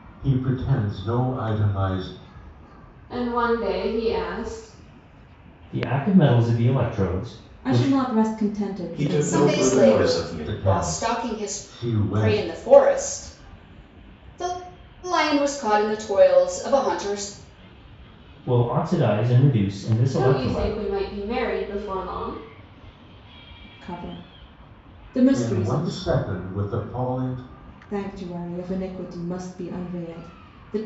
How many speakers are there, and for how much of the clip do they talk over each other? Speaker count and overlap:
6, about 16%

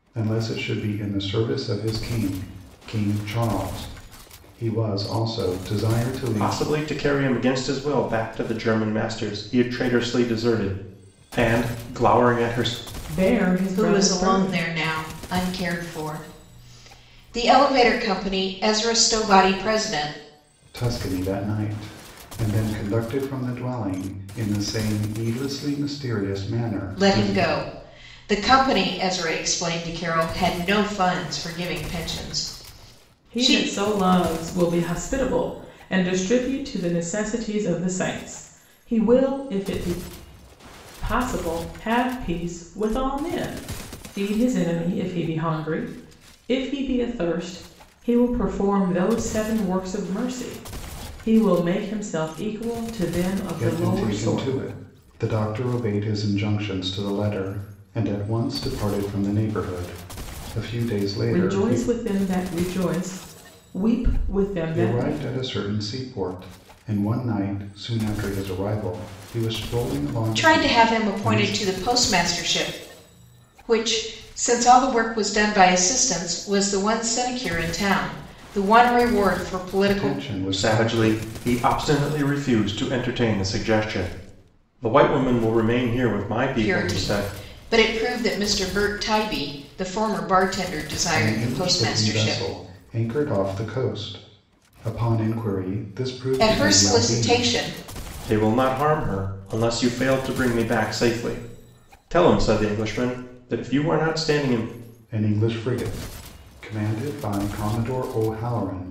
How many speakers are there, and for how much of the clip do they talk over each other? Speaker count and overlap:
4, about 9%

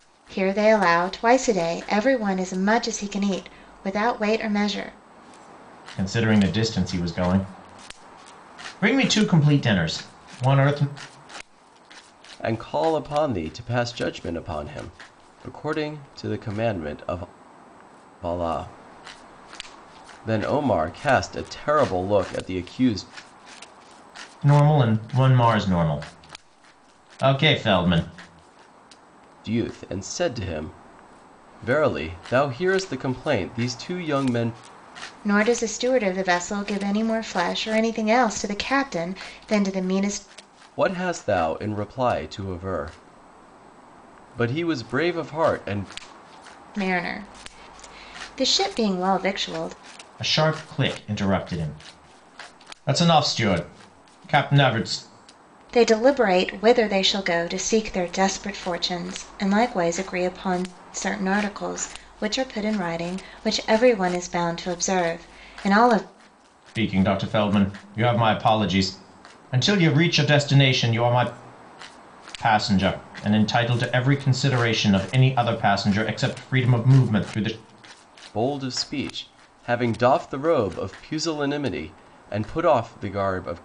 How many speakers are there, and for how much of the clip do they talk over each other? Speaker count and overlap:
3, no overlap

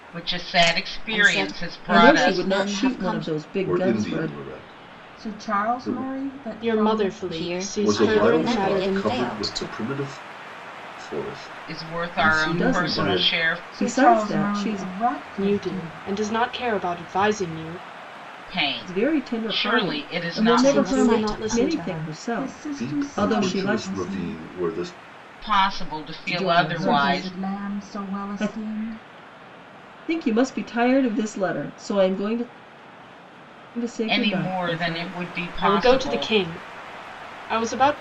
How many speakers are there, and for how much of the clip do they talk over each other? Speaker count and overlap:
6, about 54%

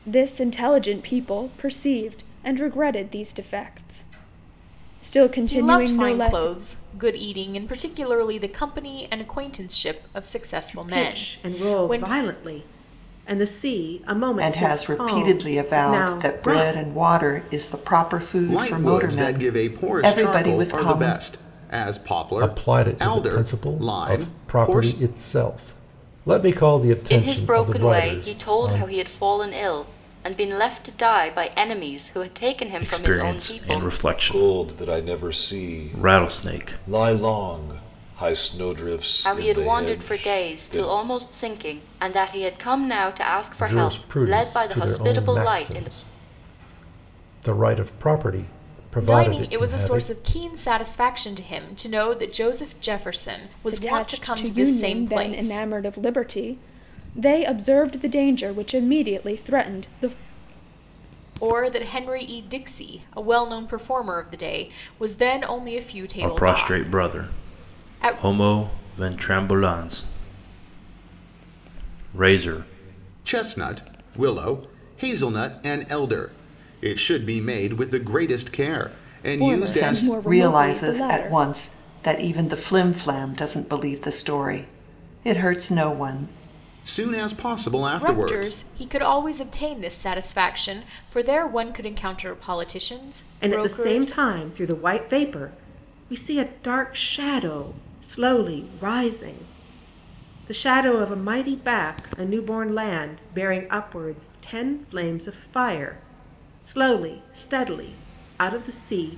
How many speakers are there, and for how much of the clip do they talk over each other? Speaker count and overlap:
9, about 27%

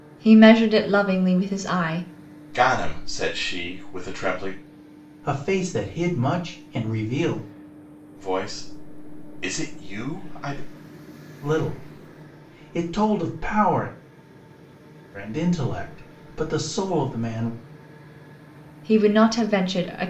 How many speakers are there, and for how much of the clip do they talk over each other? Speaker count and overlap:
3, no overlap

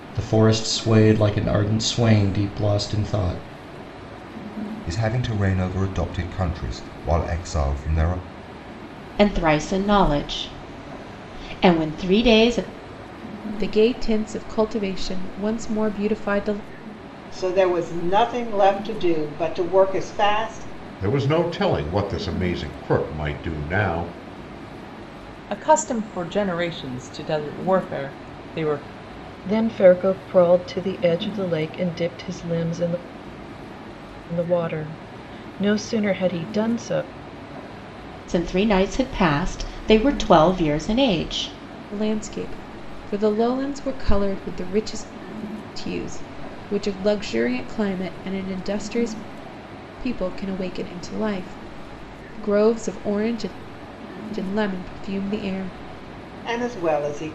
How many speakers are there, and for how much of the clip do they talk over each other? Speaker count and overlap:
8, no overlap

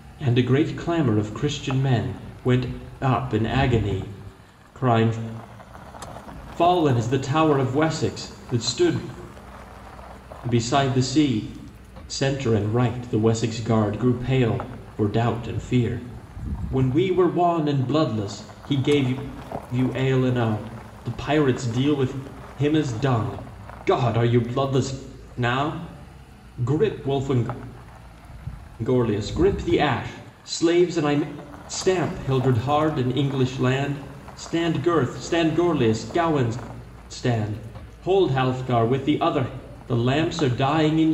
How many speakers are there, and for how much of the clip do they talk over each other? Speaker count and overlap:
1, no overlap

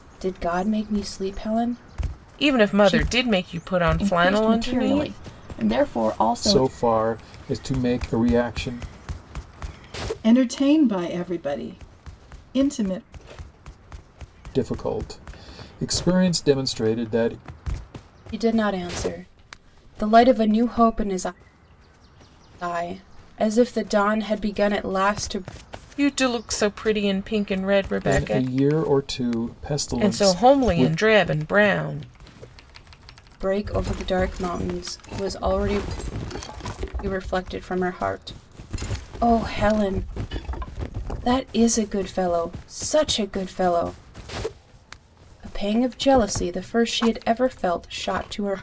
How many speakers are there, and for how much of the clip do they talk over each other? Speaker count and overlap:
5, about 8%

